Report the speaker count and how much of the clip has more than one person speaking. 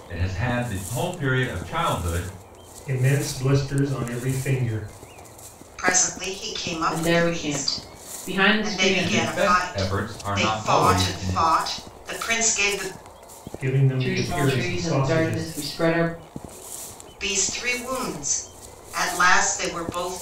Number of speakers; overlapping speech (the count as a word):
four, about 26%